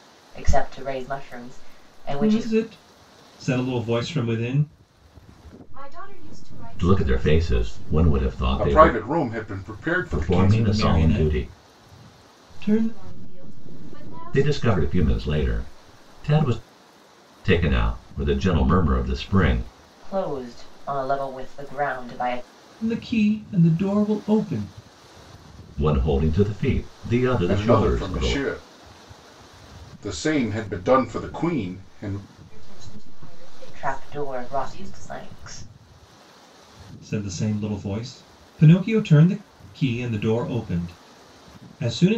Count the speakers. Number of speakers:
5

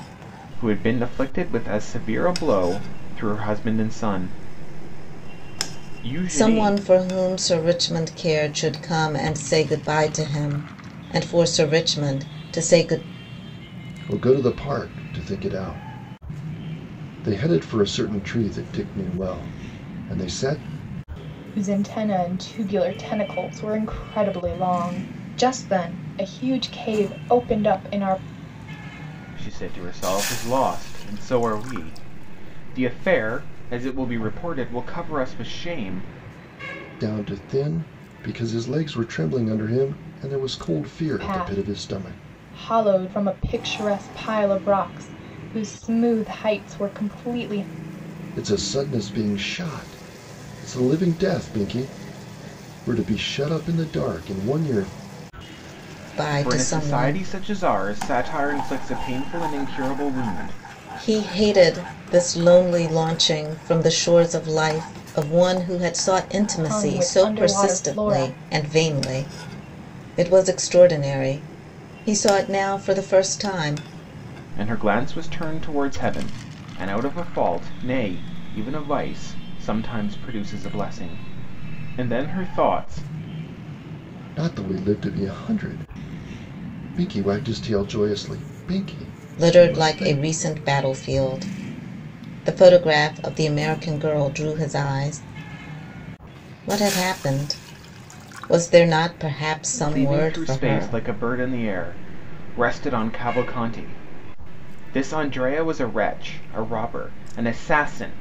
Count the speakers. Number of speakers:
4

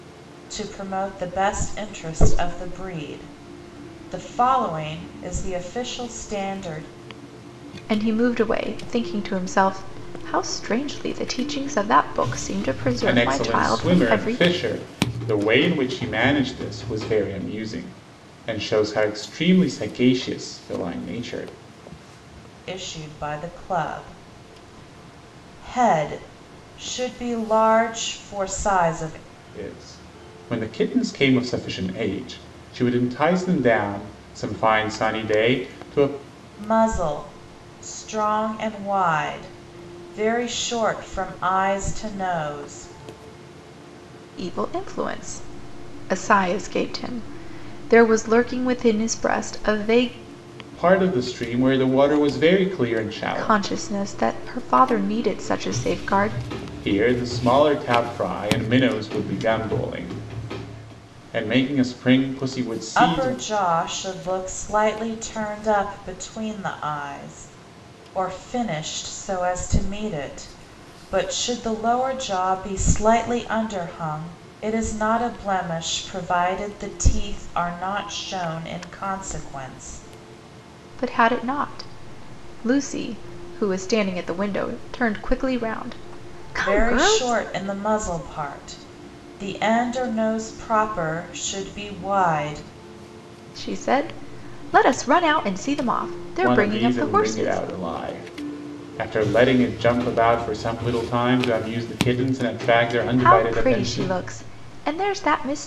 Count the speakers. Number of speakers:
3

